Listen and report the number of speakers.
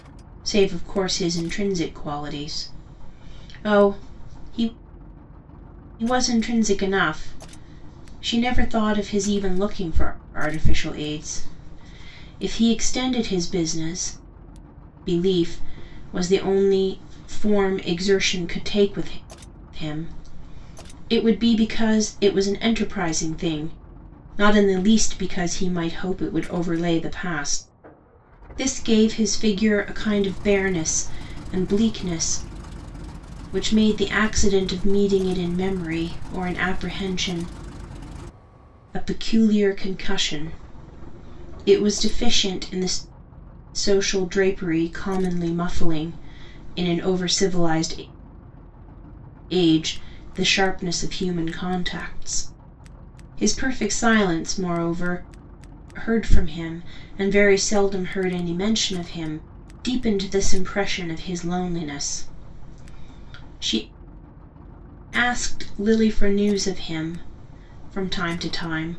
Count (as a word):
one